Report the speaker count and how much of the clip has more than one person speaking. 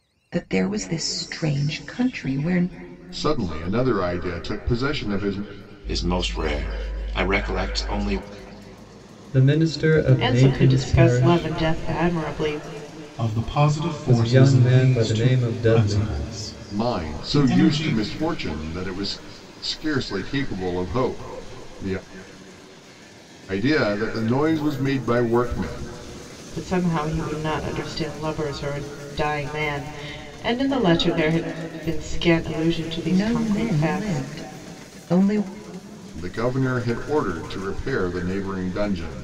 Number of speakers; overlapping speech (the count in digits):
6, about 14%